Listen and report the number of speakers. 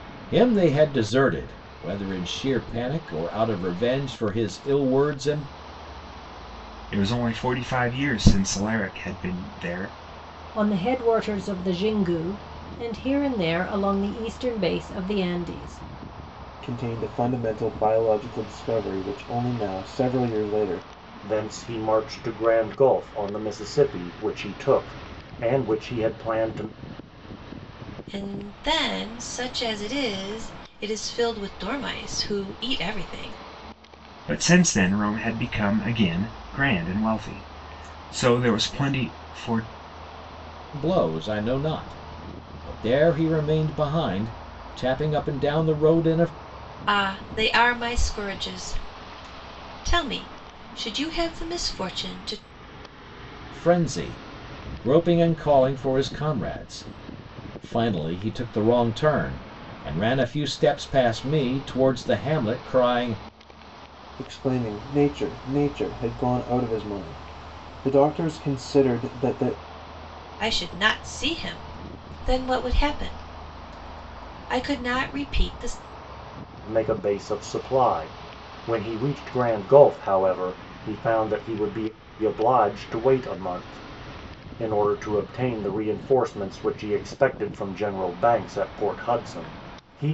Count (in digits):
6